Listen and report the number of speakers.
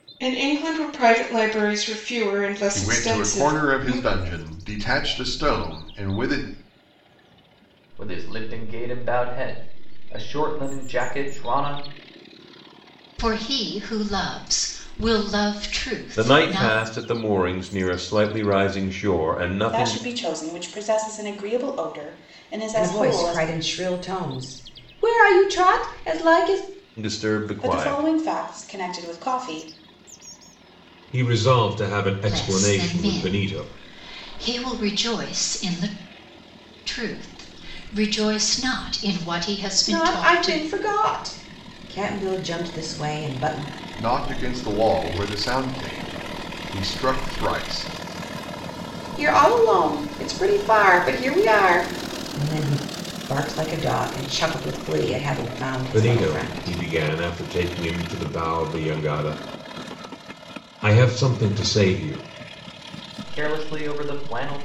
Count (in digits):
7